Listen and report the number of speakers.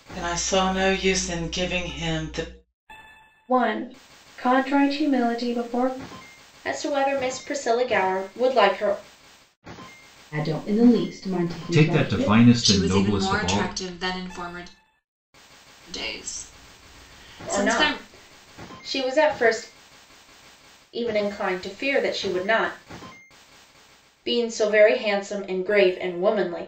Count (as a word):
six